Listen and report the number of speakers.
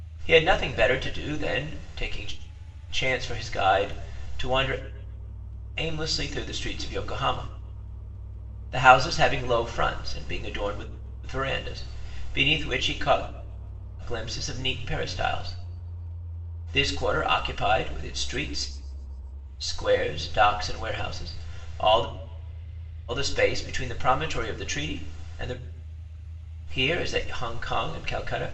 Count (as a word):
one